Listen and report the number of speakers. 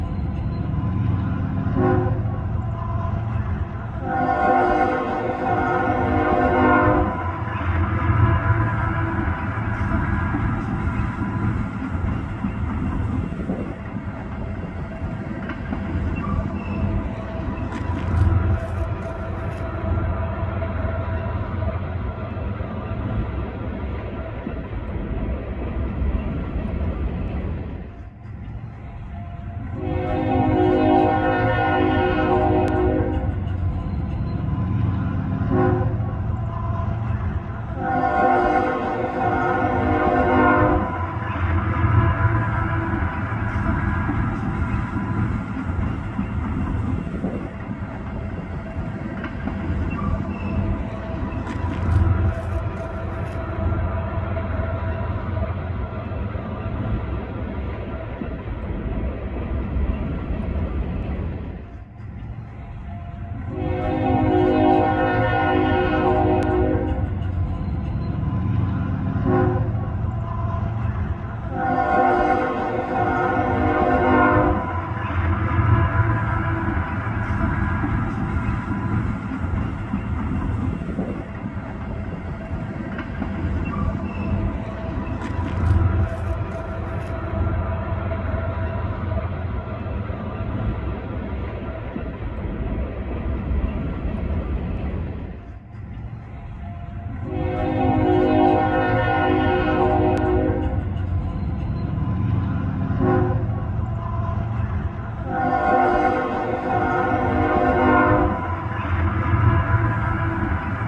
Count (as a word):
zero